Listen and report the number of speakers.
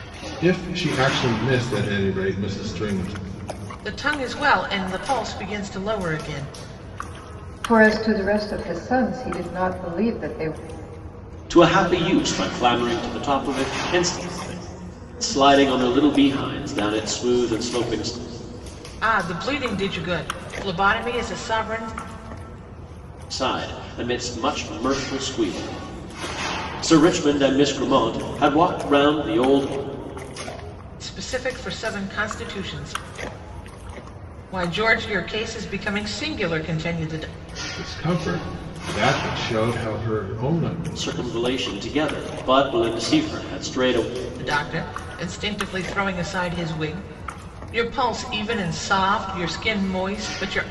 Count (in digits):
4